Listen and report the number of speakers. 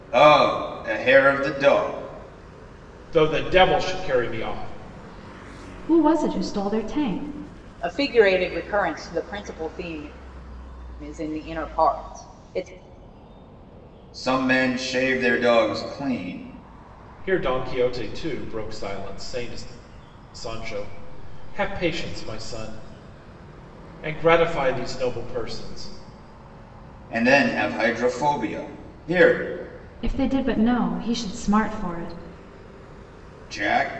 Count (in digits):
4